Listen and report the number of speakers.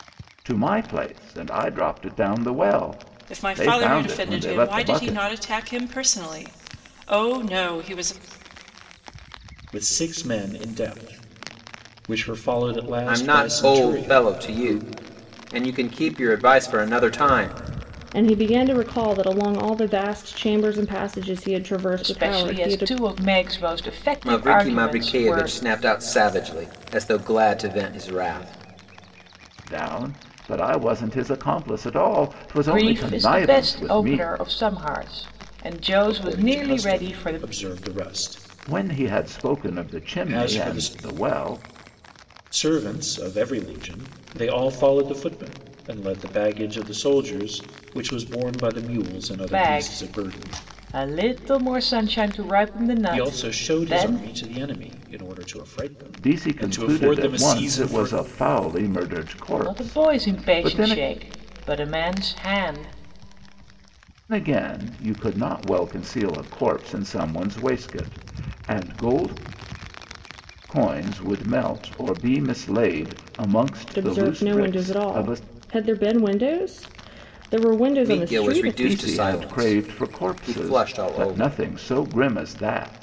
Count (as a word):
six